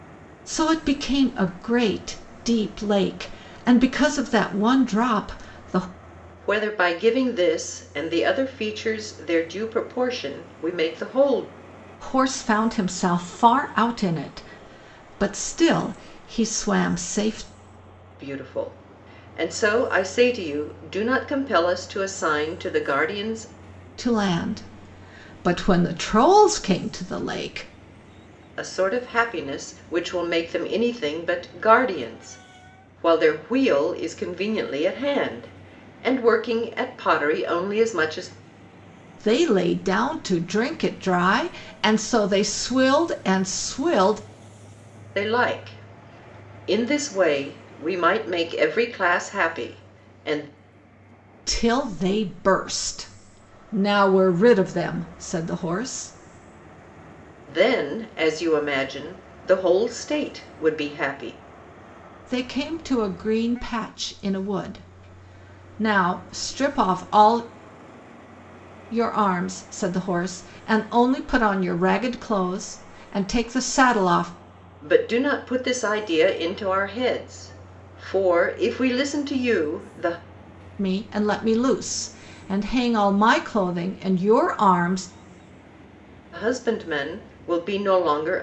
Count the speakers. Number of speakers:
2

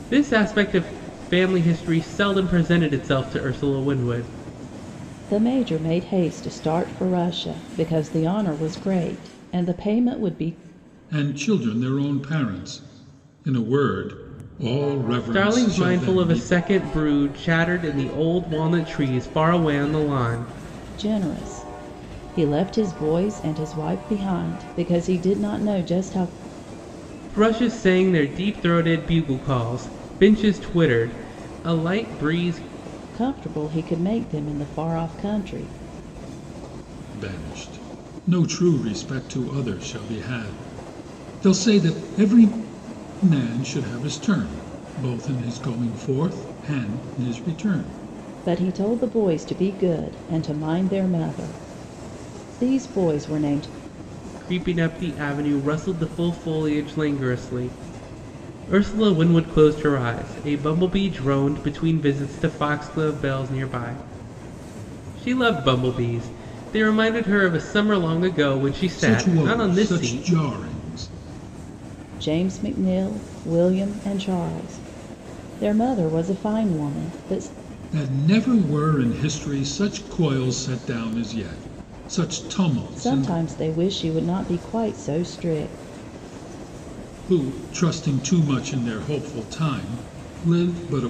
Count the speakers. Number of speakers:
3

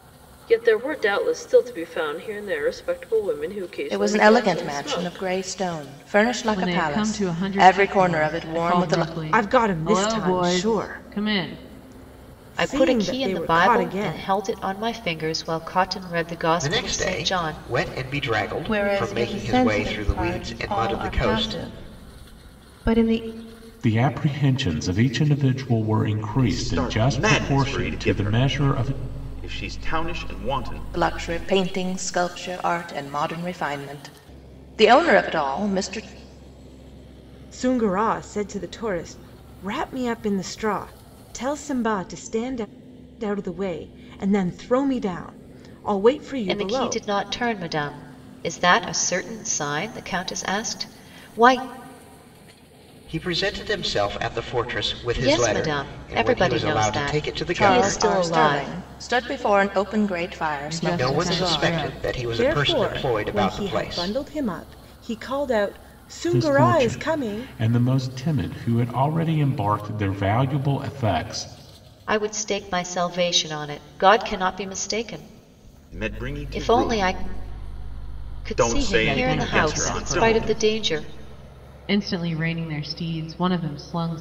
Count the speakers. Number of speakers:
9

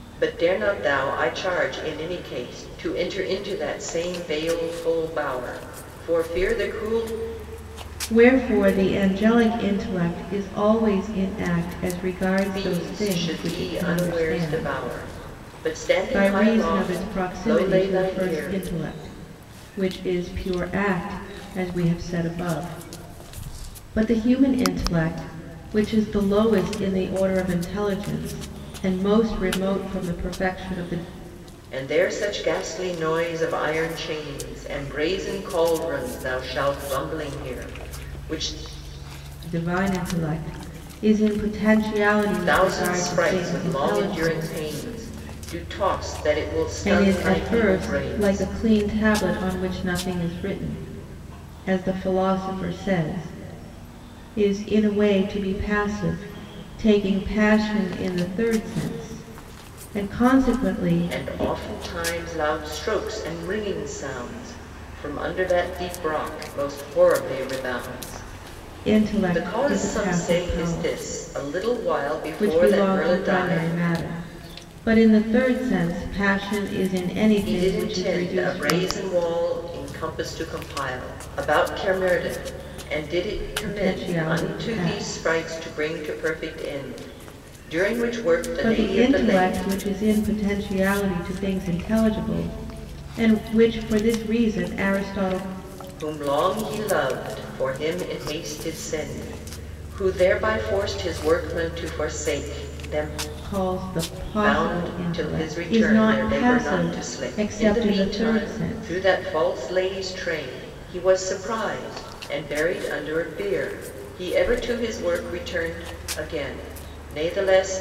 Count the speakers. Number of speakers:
2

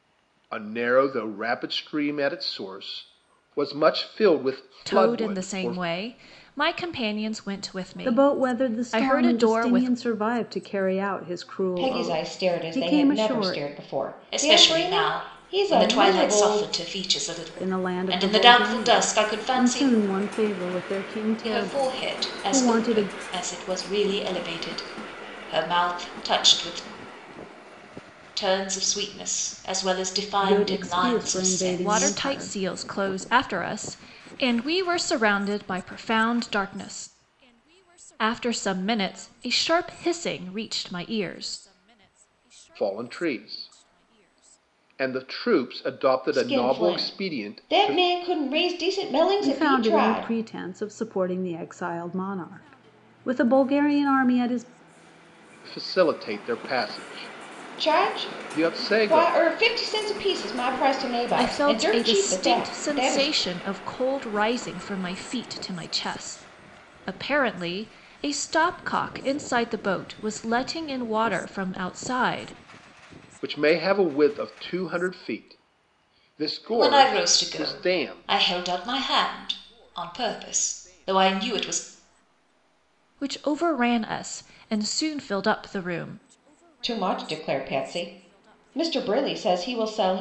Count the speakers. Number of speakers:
5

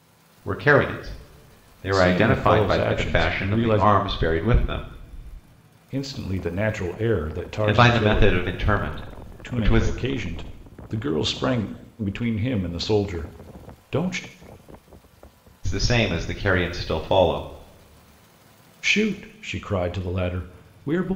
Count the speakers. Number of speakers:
2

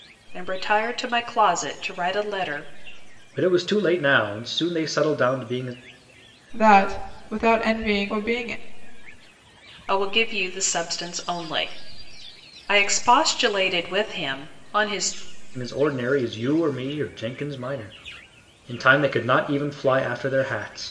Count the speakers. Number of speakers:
3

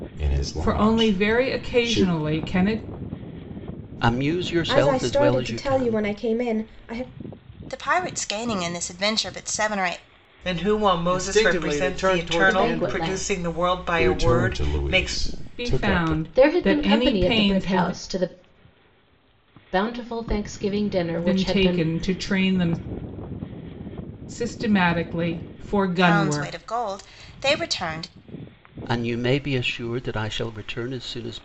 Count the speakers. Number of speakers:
8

